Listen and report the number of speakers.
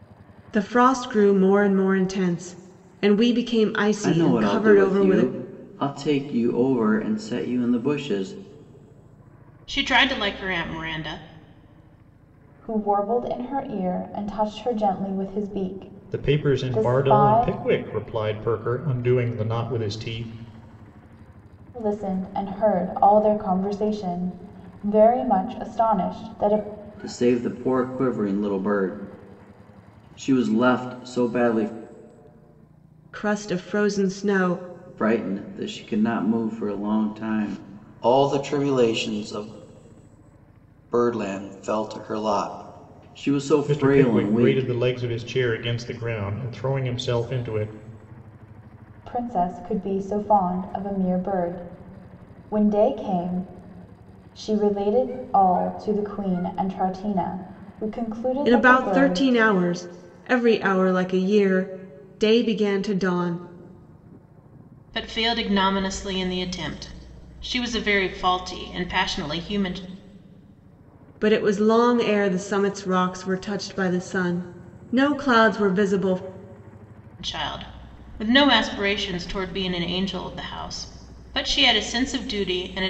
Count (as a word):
five